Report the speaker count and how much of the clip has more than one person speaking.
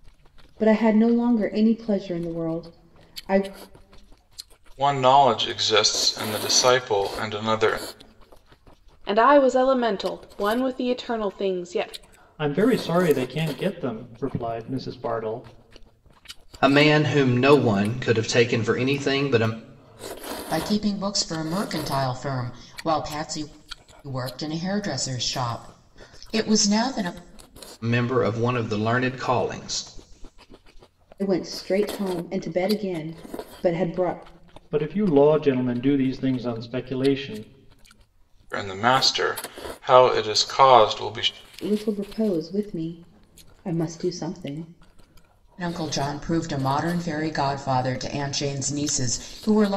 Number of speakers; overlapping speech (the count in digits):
6, no overlap